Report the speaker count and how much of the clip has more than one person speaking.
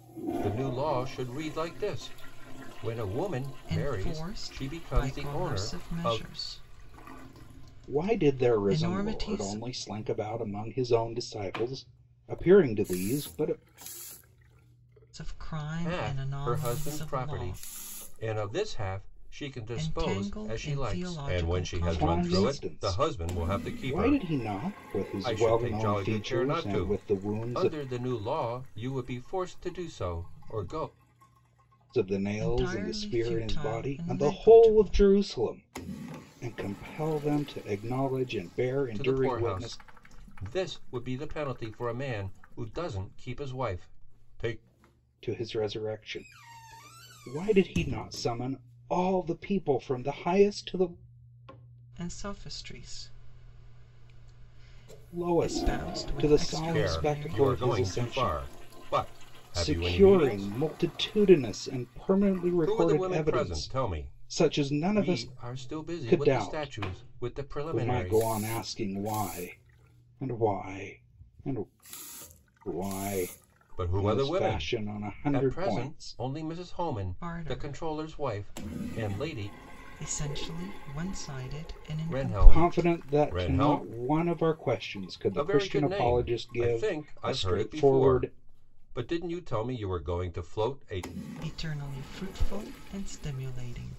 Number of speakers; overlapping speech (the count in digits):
3, about 38%